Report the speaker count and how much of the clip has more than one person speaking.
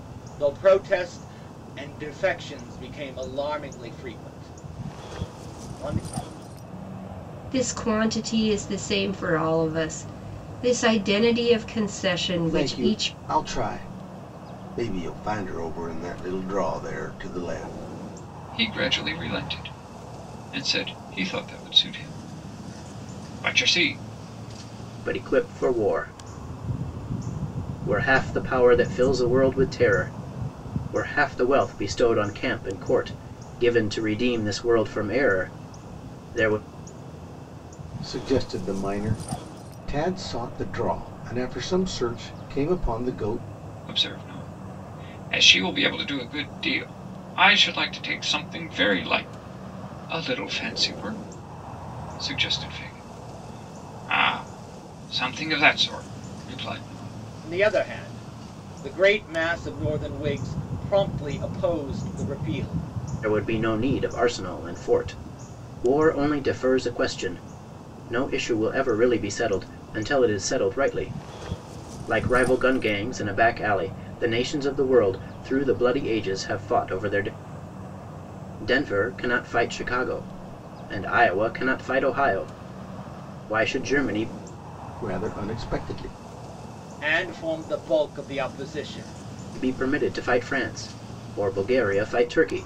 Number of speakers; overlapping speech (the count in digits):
5, about 1%